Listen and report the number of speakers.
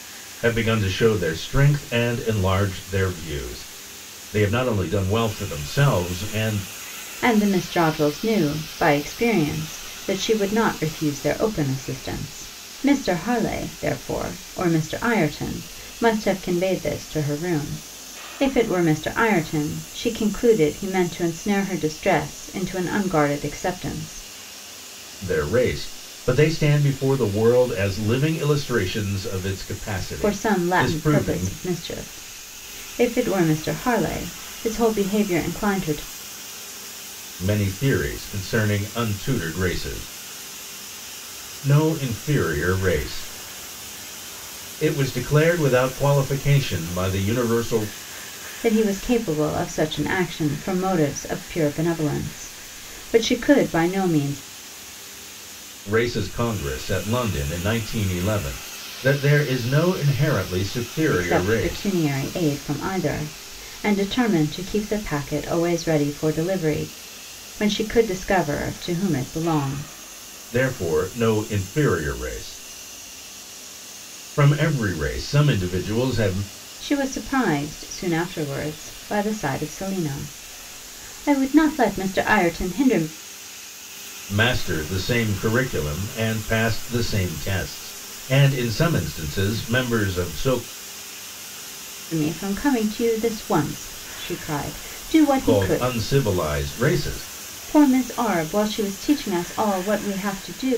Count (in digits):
2